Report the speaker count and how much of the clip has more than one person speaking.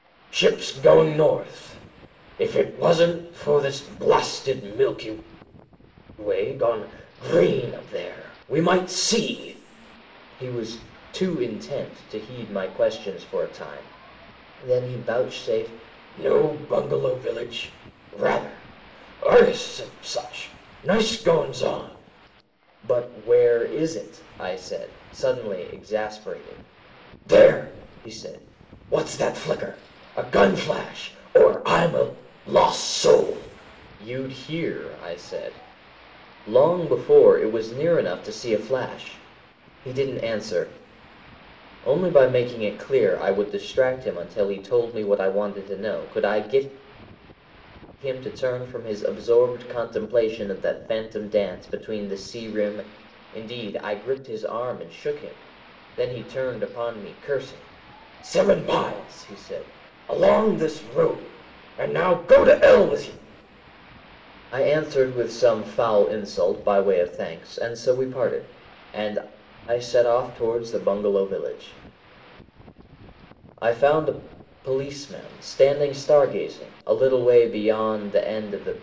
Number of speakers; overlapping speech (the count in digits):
1, no overlap